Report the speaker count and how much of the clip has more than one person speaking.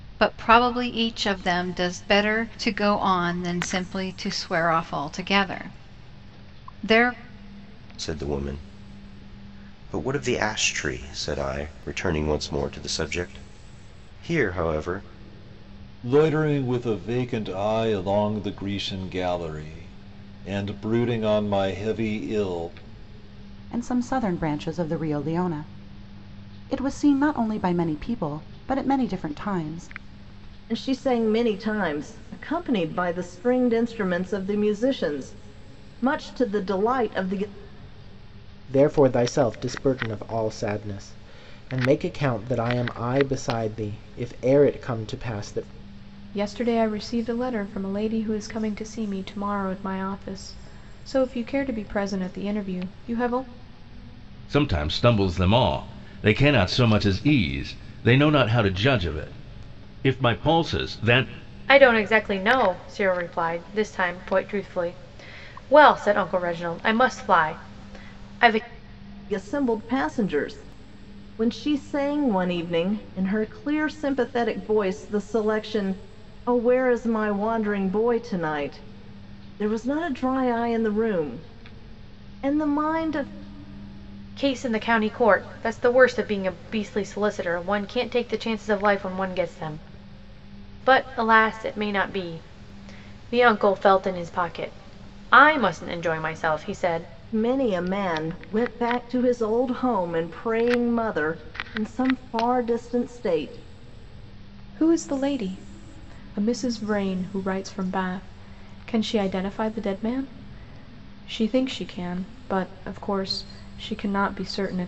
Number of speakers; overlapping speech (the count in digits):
9, no overlap